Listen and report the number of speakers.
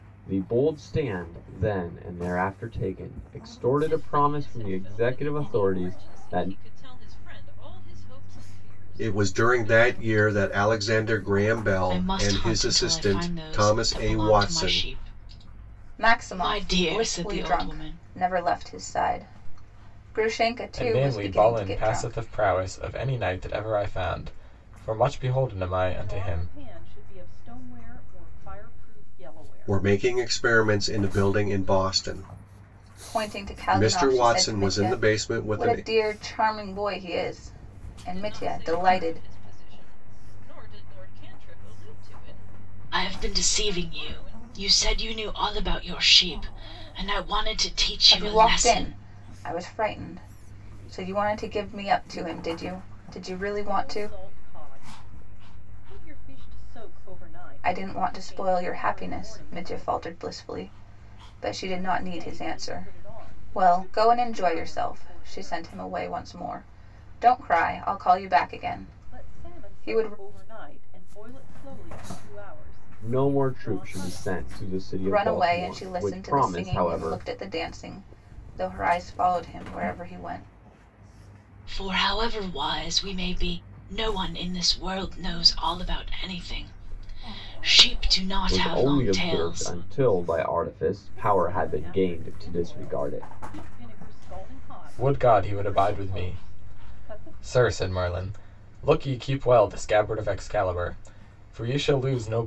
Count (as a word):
seven